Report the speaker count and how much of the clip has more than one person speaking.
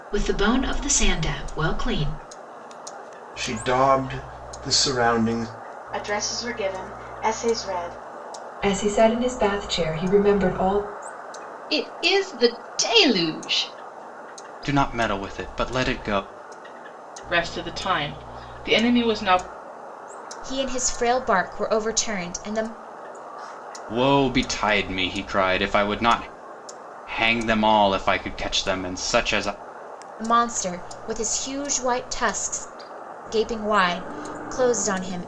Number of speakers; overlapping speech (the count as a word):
eight, no overlap